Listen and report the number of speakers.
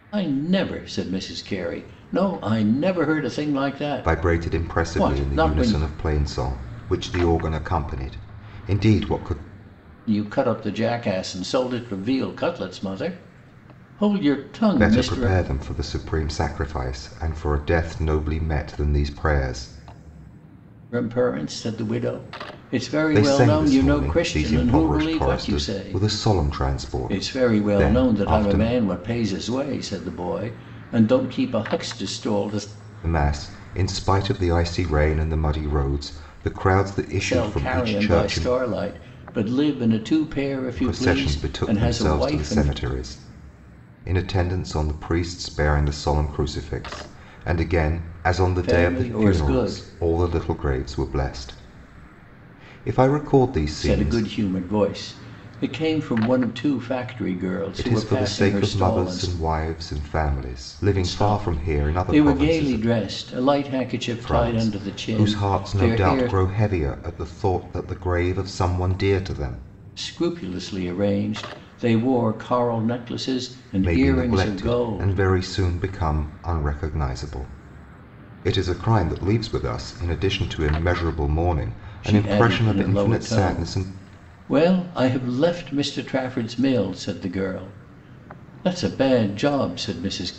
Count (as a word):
two